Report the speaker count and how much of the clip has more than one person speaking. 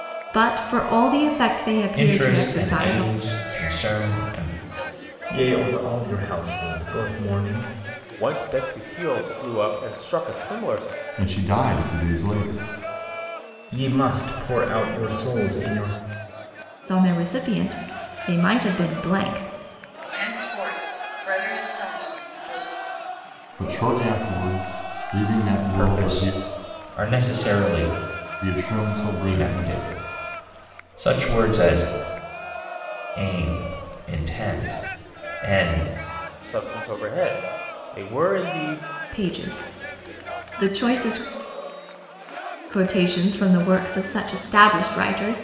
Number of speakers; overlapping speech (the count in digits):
6, about 8%